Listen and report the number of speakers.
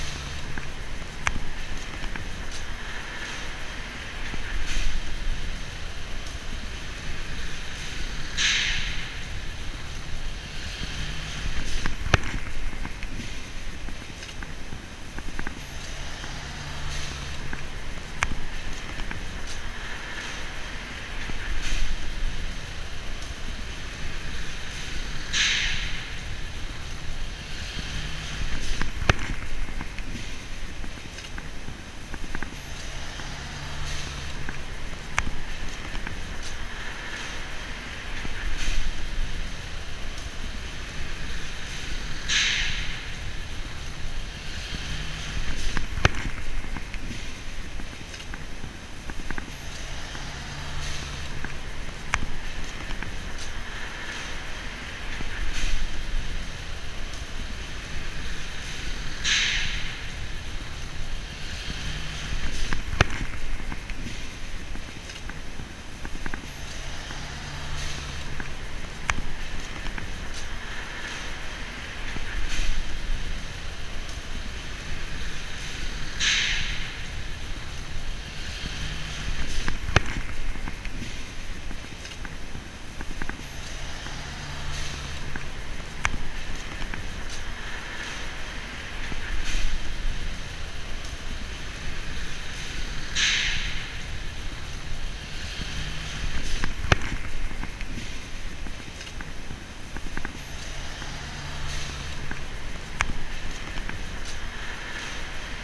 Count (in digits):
0